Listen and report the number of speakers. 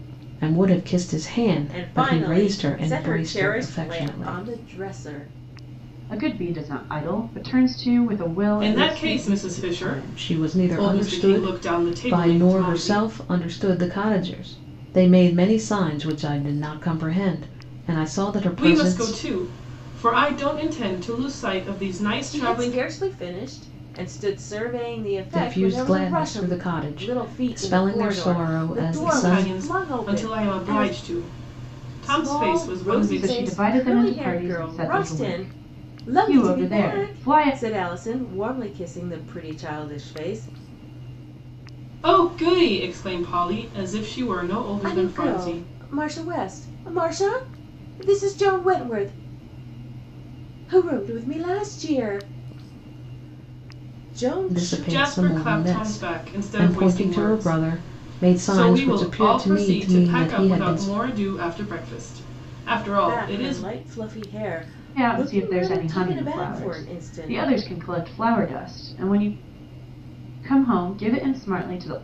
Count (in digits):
4